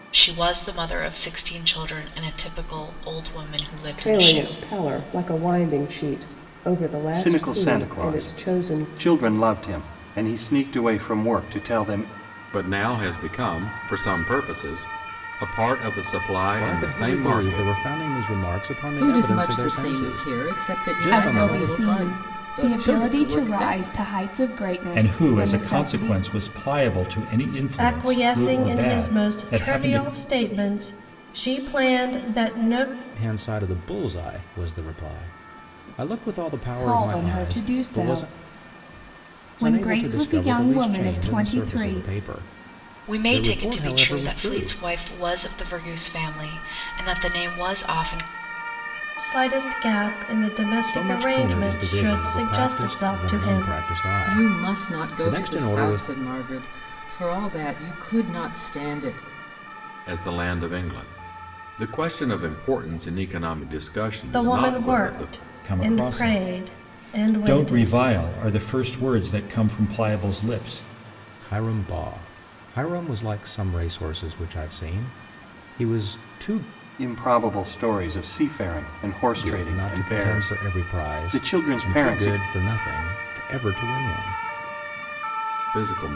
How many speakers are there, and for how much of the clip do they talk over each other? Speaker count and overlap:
nine, about 34%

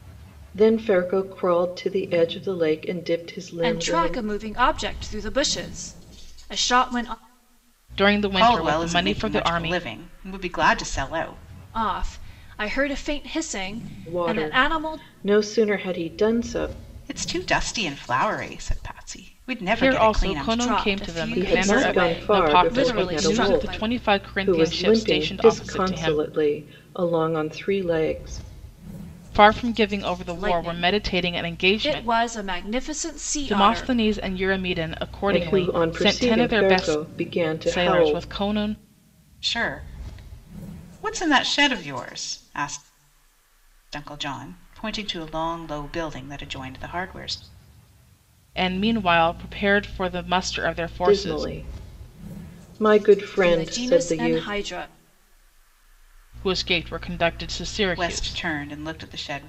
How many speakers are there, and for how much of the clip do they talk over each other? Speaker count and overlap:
four, about 28%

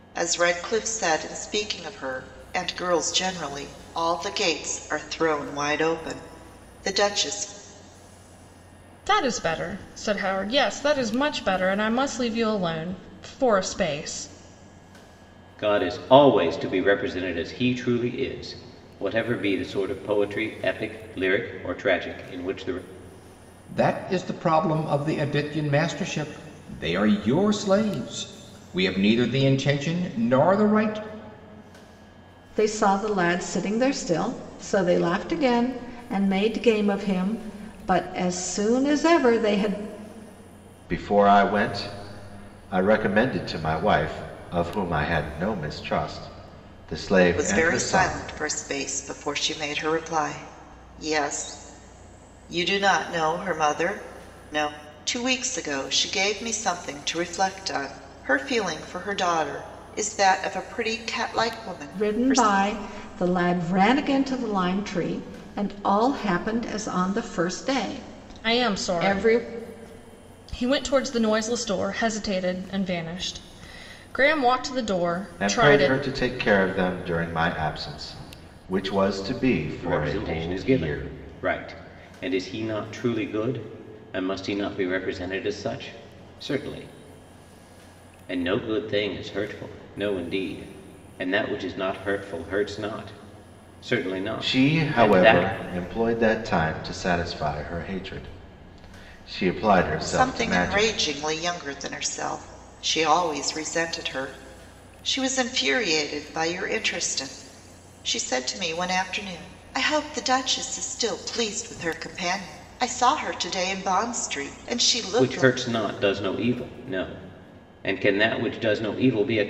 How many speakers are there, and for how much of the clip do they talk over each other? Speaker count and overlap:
six, about 6%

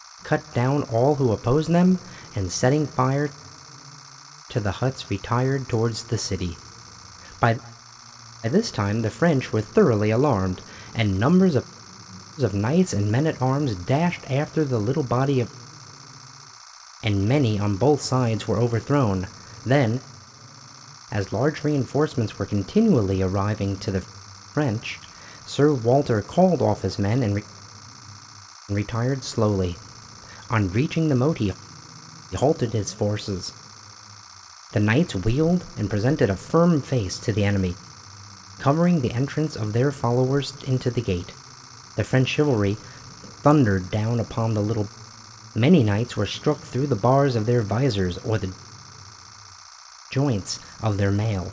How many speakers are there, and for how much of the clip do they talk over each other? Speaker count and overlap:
one, no overlap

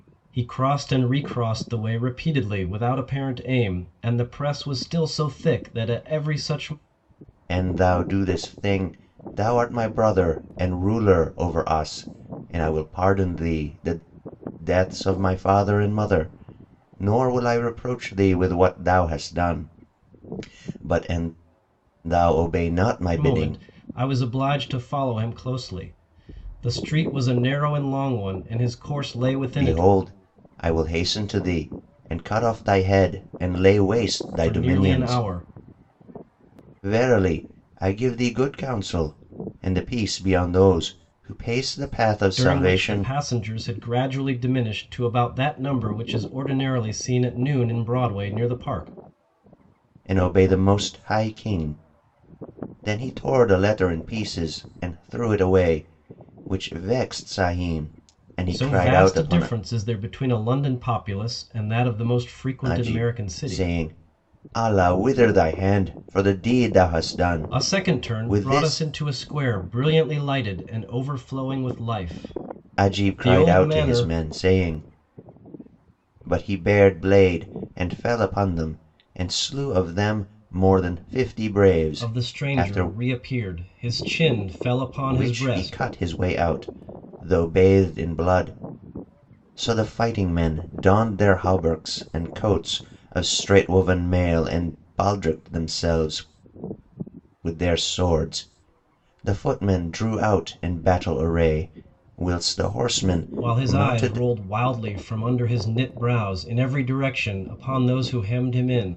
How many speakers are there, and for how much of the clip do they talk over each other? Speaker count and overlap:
two, about 9%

